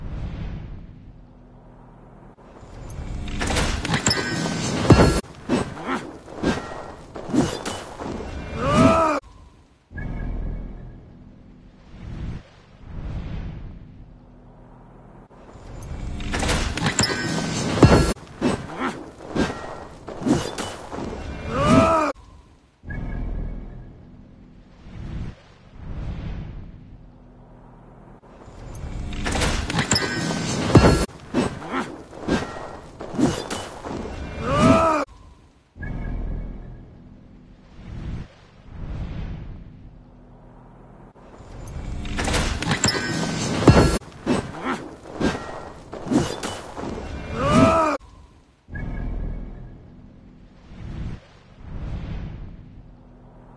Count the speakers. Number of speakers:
0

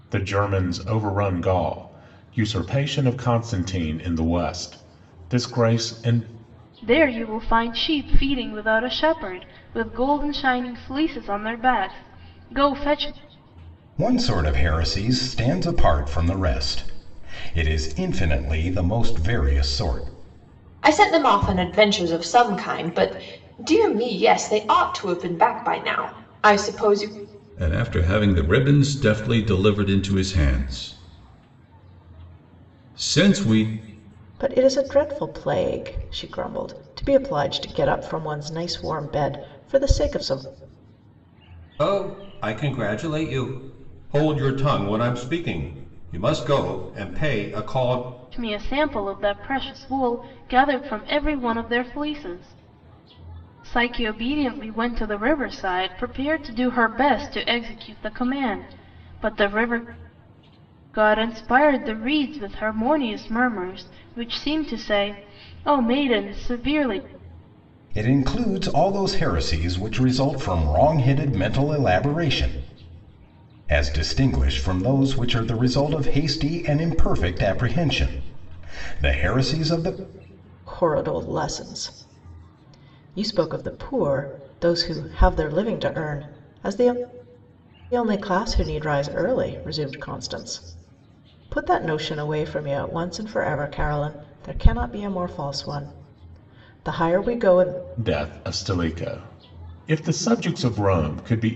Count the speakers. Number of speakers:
7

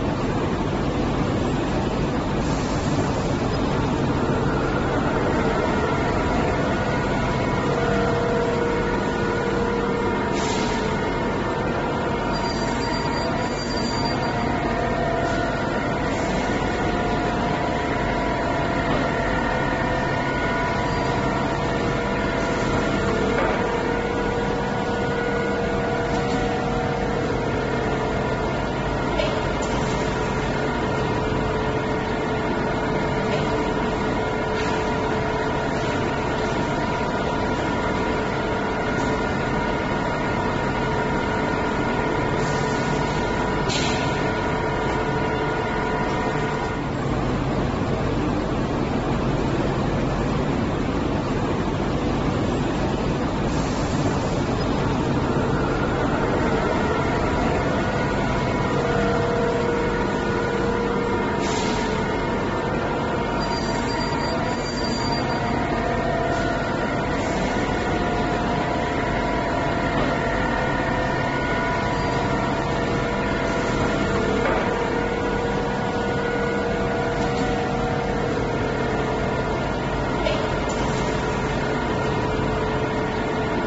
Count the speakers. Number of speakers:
0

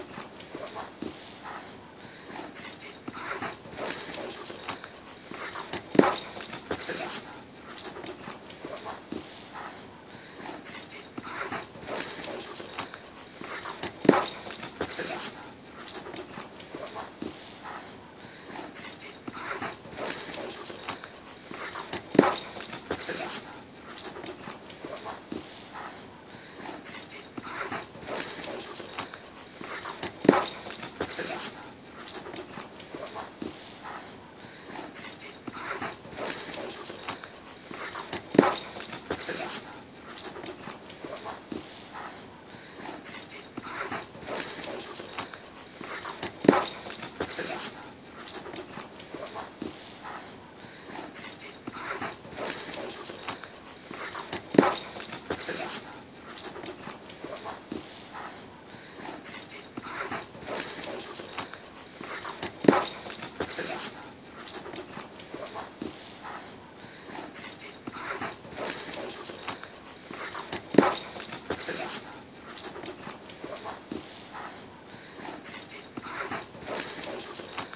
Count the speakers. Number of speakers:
0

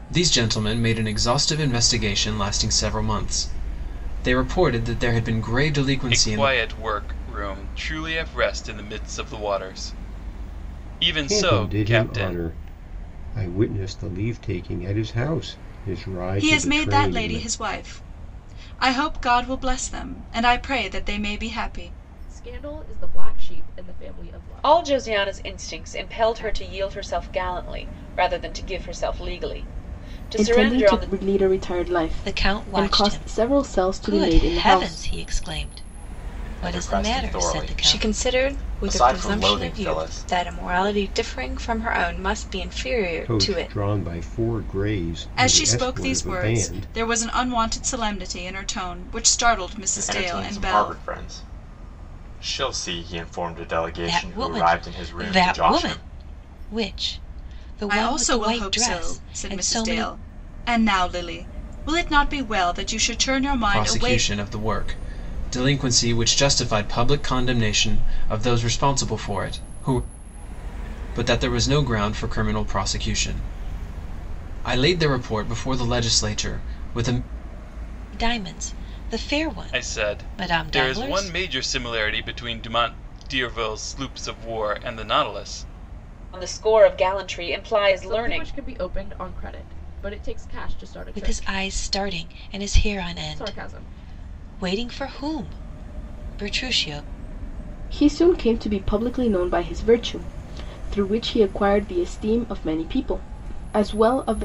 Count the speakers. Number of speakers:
10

